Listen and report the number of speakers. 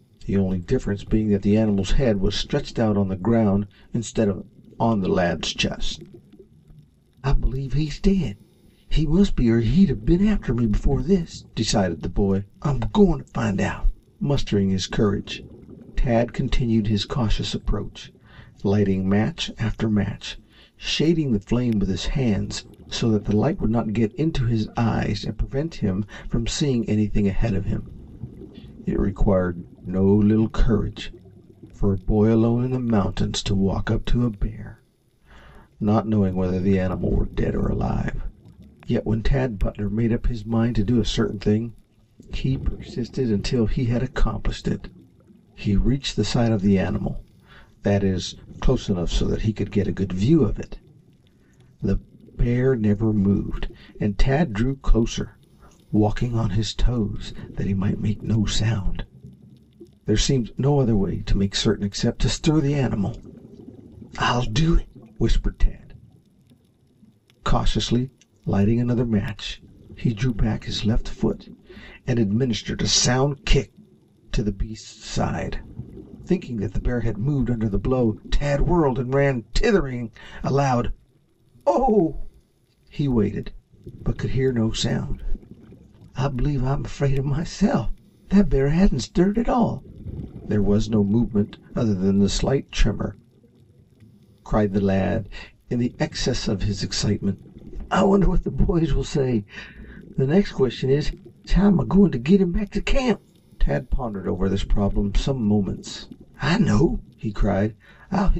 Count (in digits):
1